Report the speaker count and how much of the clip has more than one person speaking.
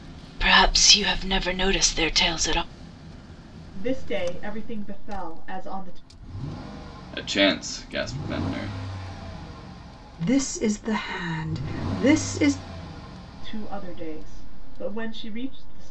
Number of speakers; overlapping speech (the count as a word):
four, no overlap